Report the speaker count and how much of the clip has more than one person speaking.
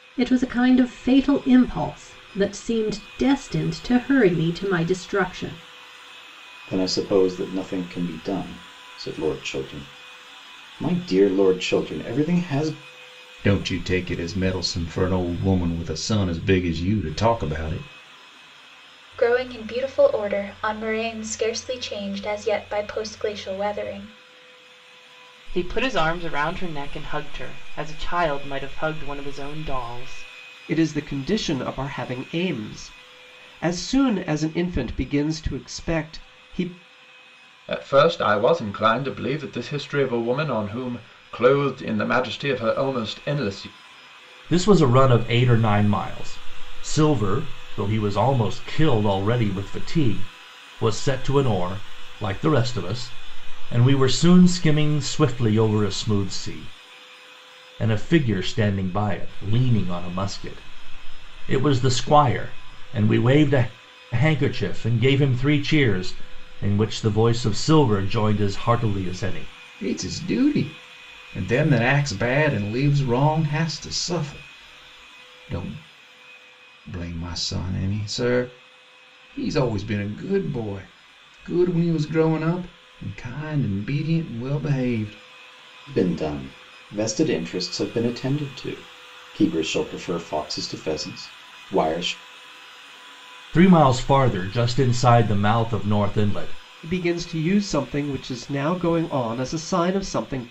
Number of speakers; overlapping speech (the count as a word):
eight, no overlap